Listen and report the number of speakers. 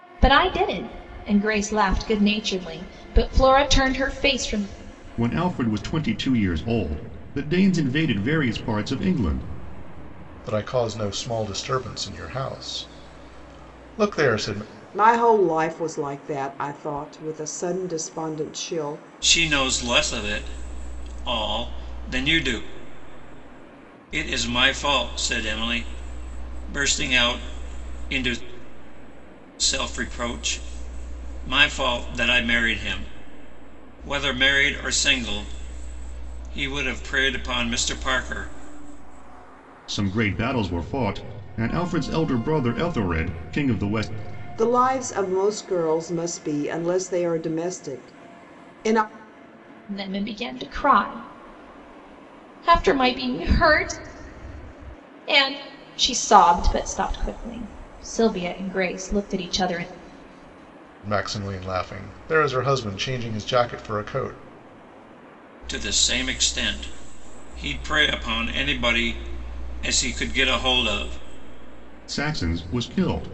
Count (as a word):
five